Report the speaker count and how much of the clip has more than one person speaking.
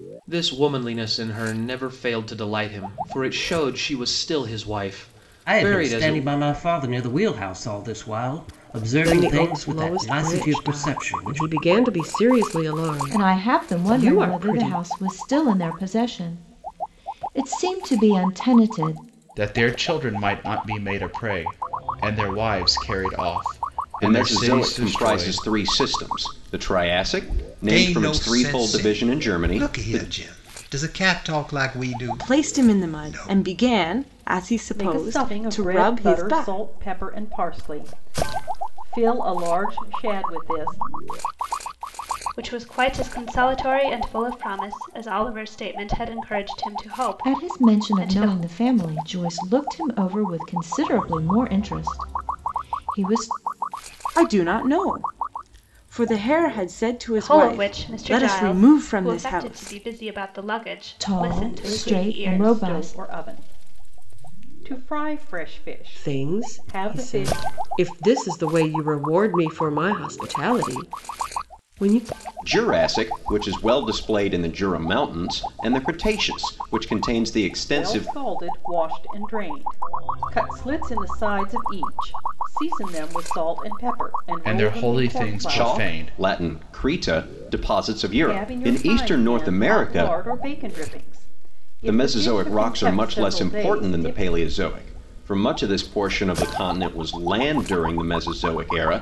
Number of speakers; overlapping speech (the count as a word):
ten, about 27%